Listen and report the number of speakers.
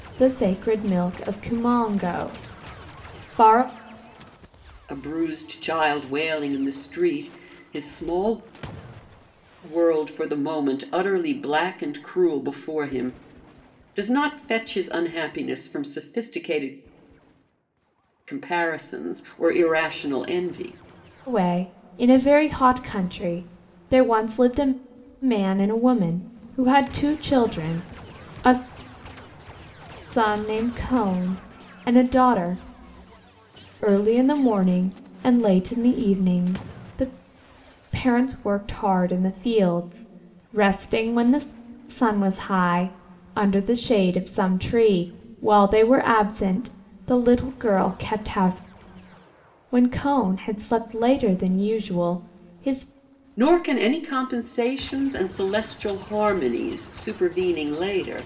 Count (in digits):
2